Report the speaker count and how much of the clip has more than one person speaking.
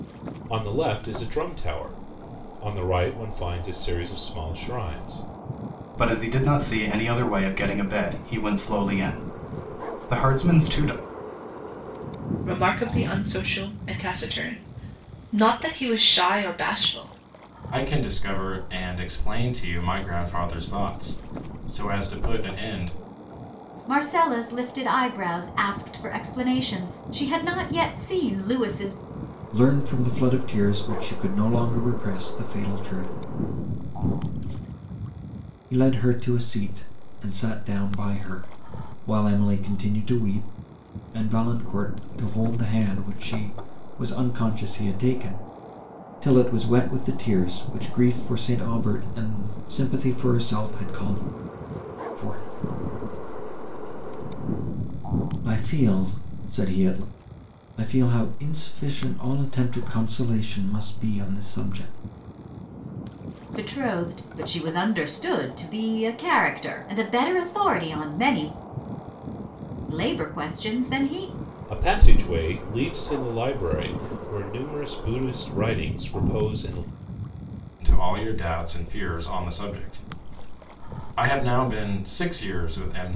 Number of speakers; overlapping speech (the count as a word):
six, no overlap